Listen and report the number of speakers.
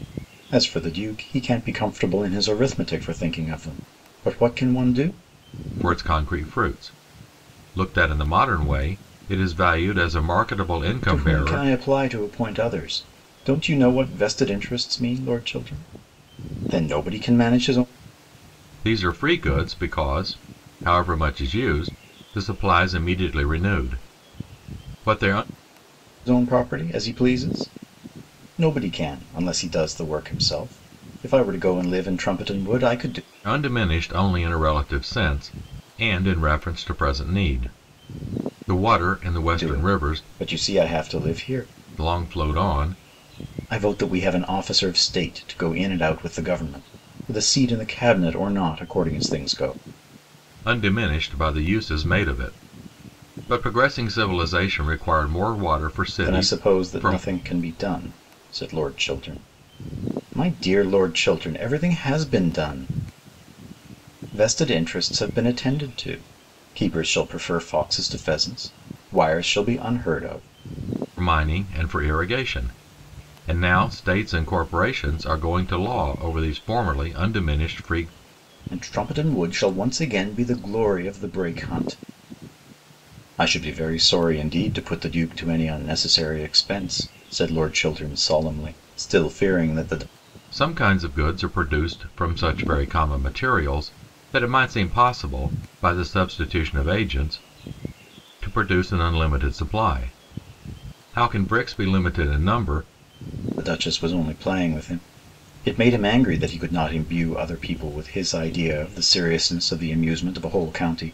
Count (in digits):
2